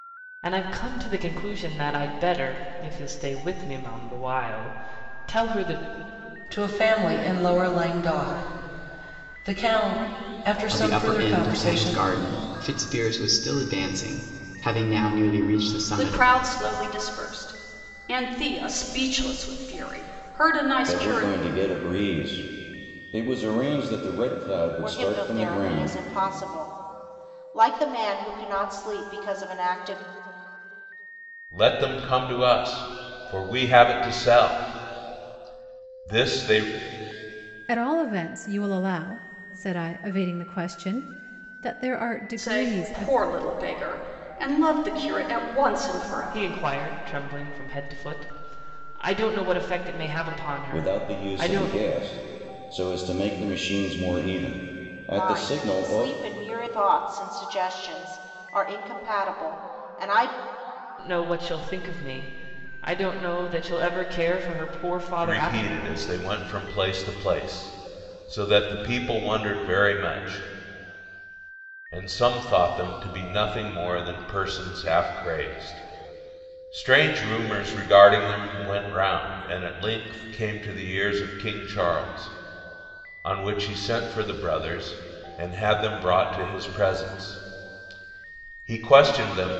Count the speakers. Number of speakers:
8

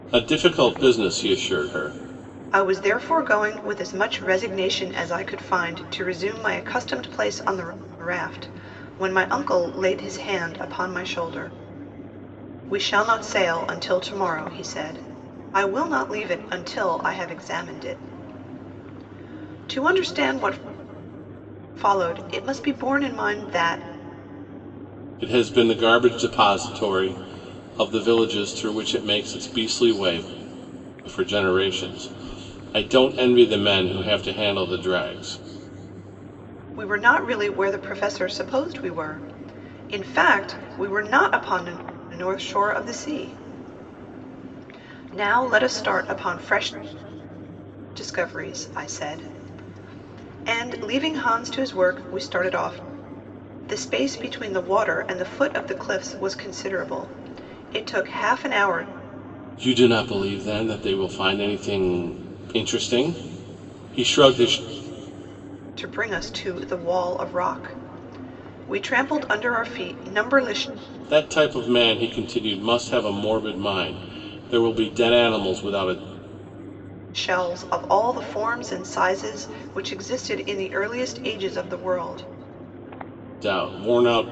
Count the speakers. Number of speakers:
2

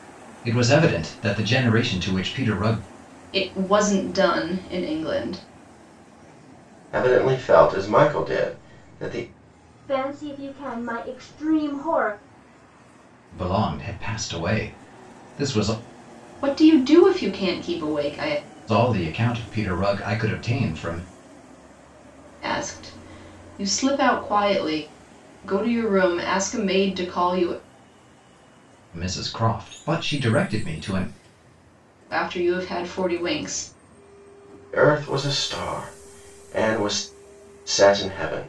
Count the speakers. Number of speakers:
4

